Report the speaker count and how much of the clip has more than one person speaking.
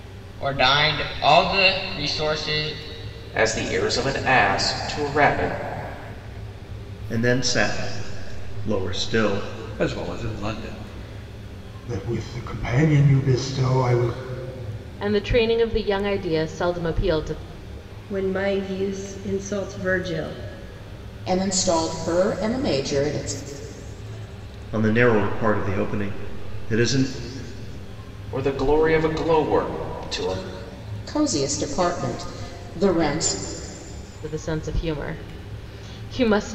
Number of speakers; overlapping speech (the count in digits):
8, no overlap